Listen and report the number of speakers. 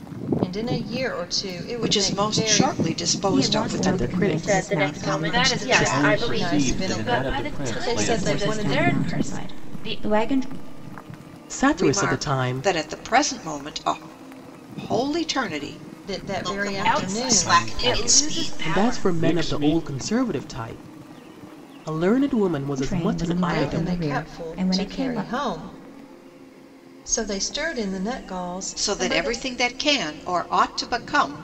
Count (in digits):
8